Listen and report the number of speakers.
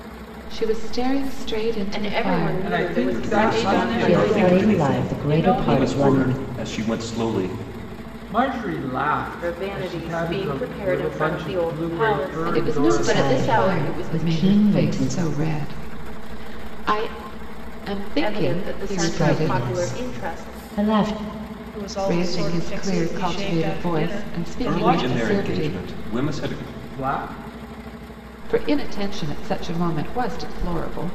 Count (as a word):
six